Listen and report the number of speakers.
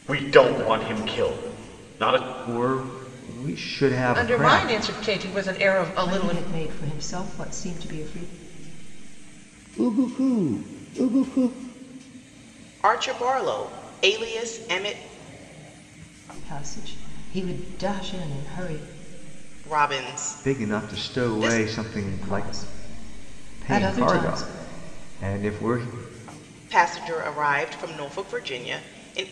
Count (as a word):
six